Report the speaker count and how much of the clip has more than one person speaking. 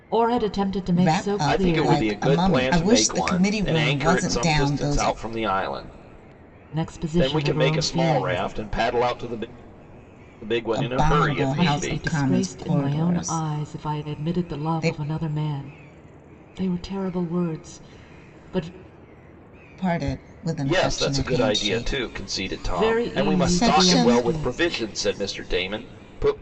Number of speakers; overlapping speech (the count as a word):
three, about 52%